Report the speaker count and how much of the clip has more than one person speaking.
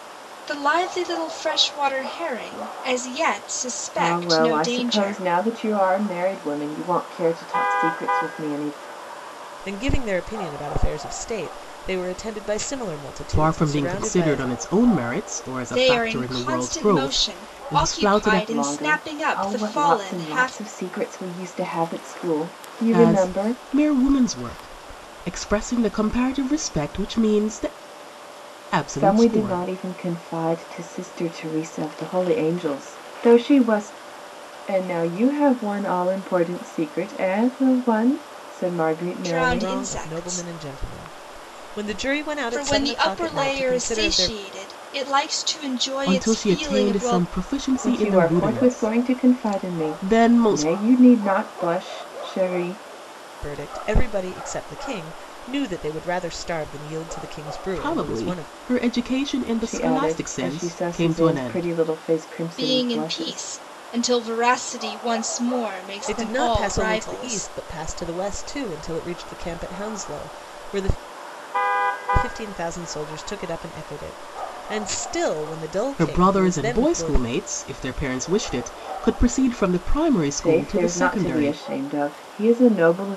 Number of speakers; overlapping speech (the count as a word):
four, about 29%